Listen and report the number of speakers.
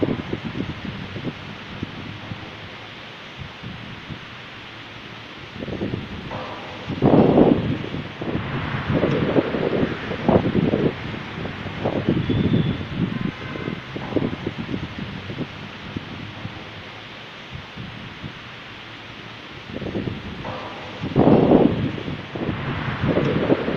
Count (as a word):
zero